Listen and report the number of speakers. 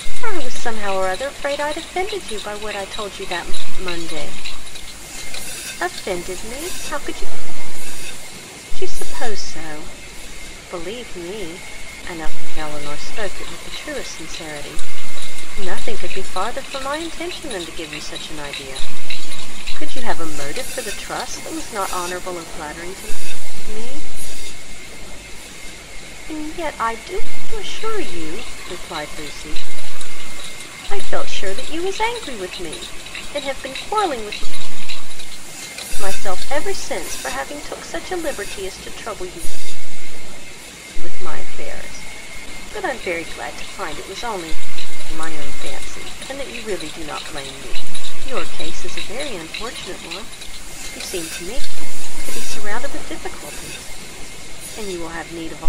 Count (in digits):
1